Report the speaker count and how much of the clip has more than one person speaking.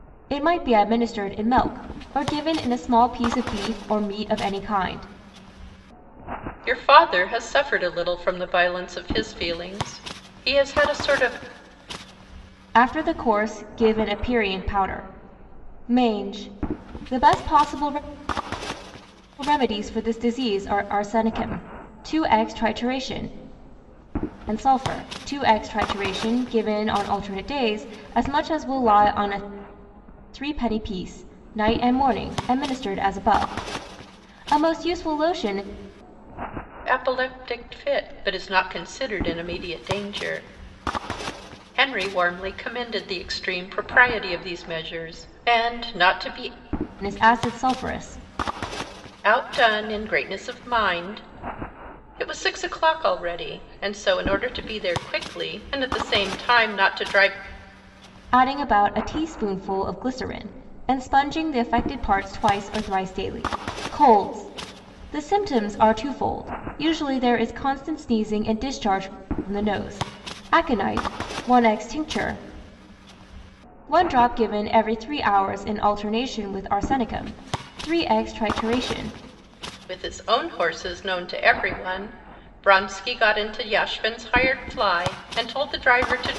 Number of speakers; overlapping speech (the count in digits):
2, no overlap